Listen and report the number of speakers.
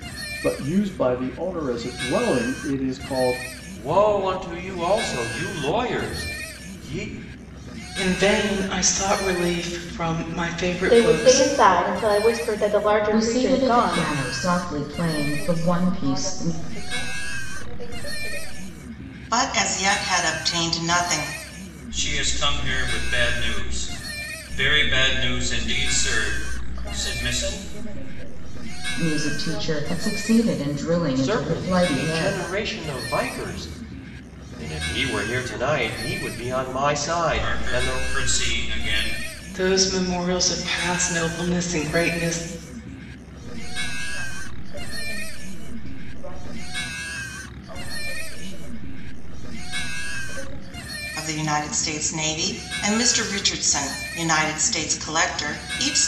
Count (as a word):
eight